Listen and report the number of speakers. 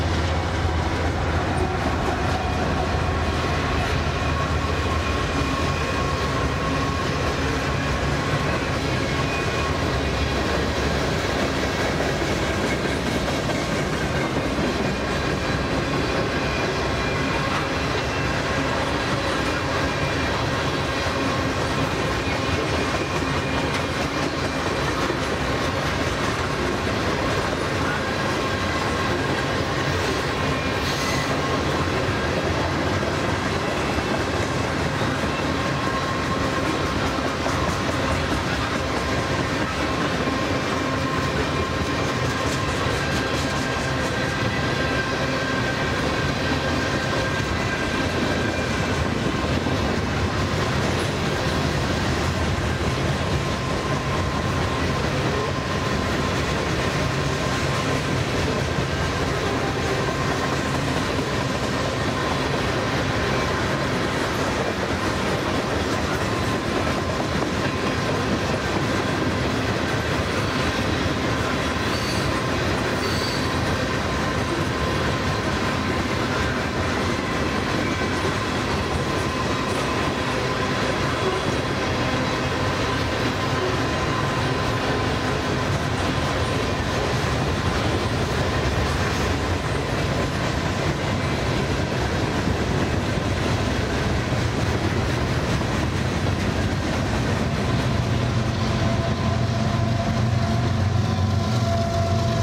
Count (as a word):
zero